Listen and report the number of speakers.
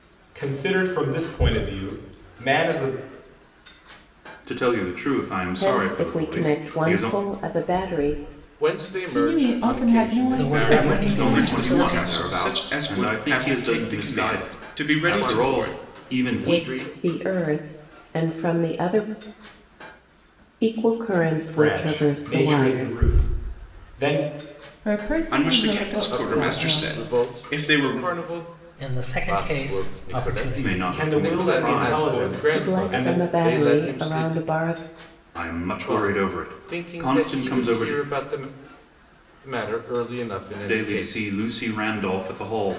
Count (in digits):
7